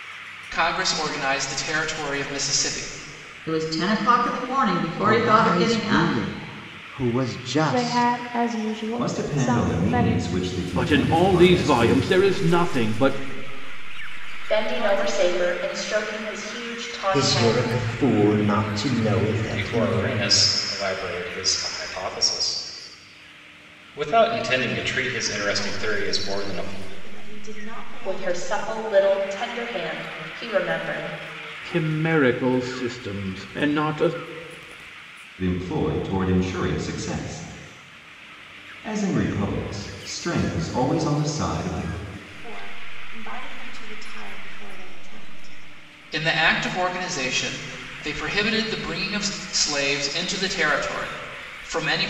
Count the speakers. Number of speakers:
10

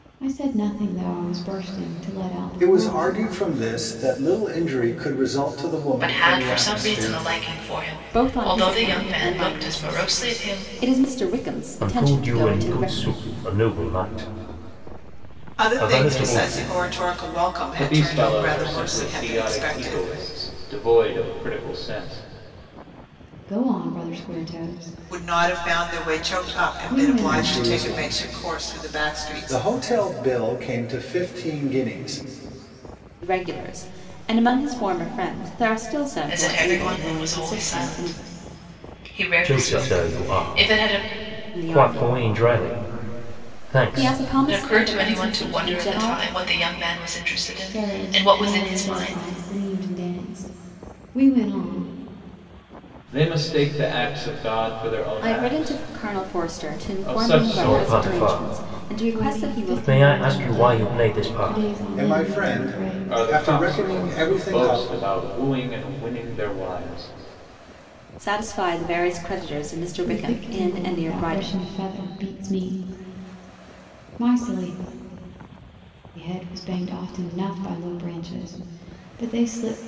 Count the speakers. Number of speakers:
7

